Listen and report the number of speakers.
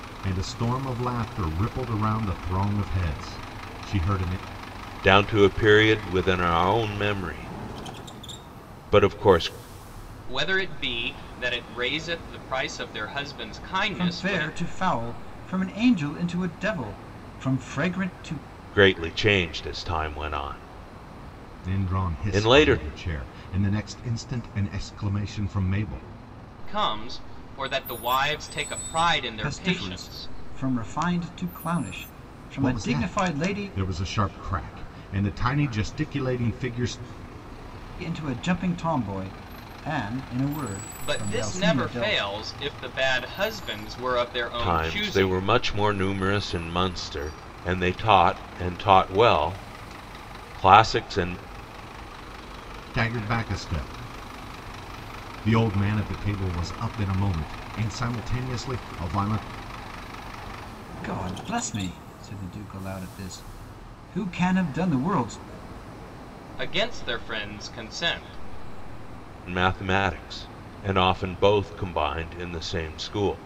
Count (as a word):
four